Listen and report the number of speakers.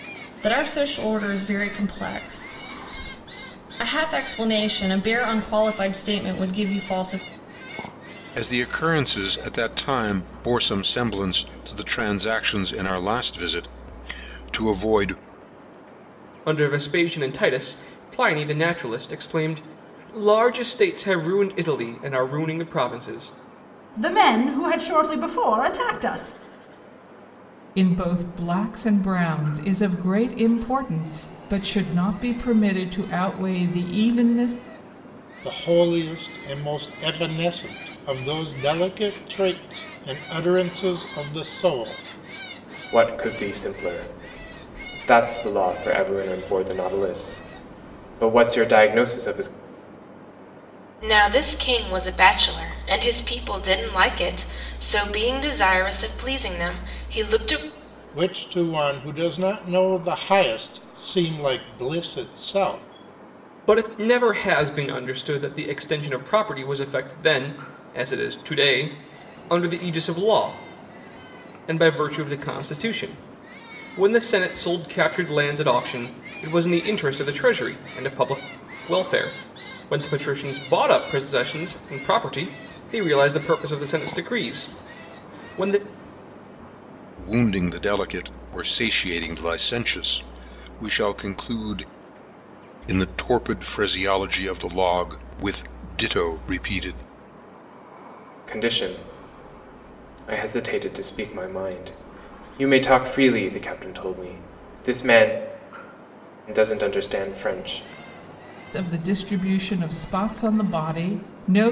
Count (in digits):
8